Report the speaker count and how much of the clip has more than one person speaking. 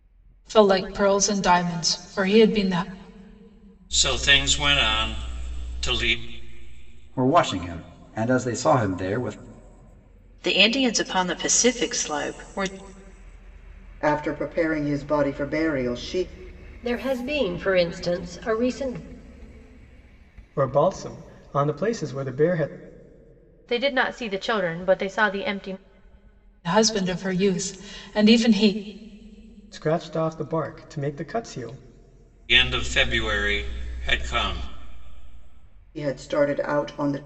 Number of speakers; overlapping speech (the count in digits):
8, no overlap